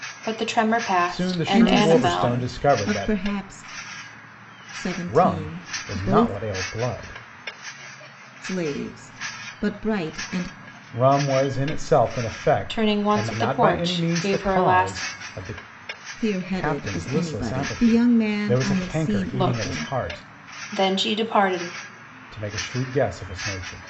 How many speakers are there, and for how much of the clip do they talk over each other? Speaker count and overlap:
three, about 39%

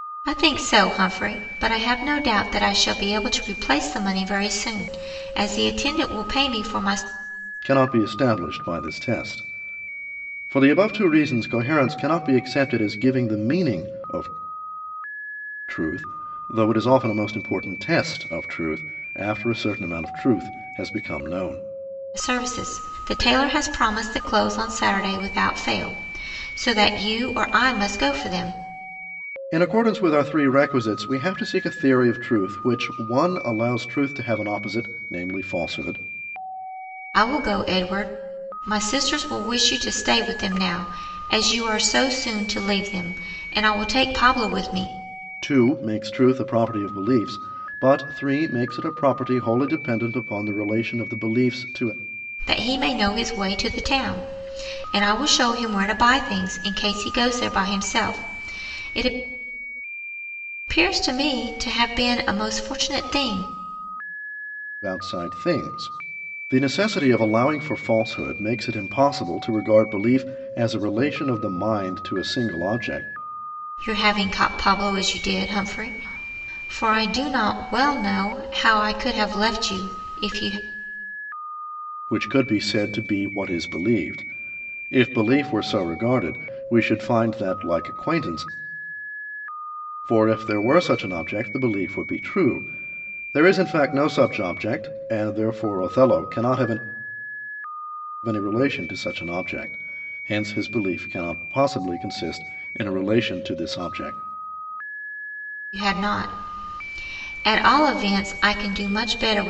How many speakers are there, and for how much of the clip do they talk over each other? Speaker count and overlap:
two, no overlap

